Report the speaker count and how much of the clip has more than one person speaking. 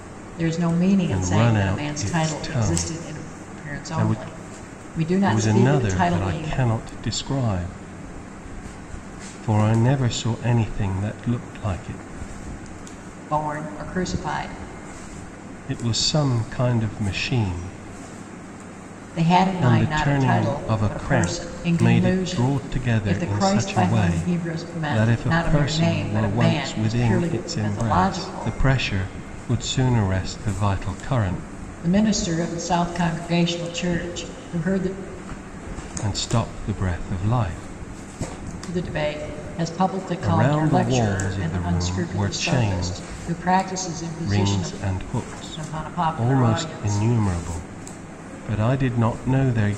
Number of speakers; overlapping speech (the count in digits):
2, about 36%